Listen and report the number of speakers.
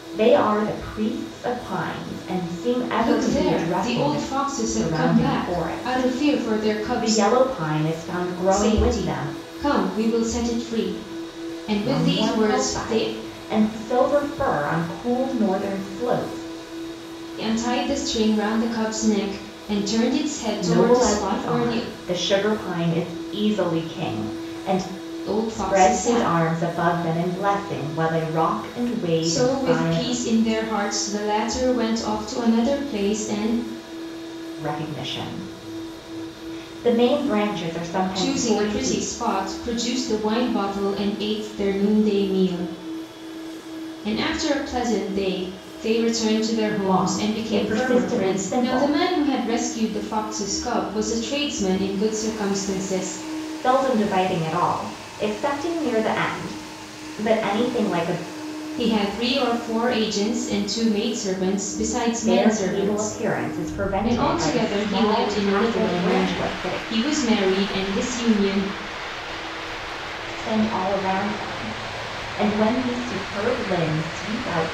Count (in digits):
2